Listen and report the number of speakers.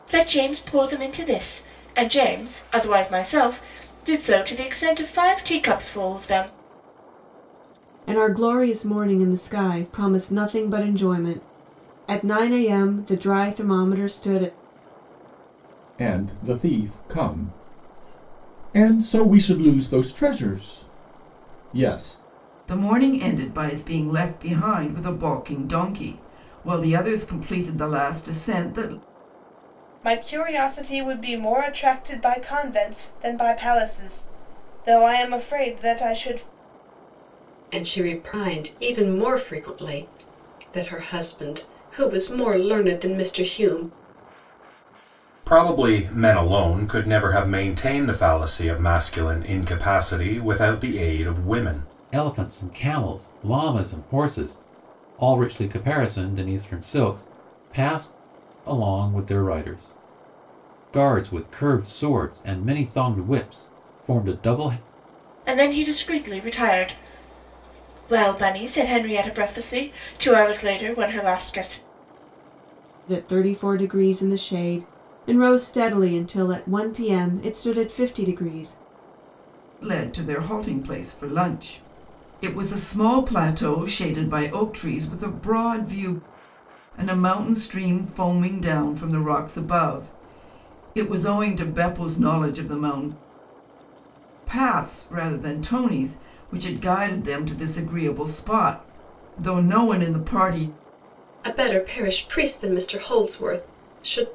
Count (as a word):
eight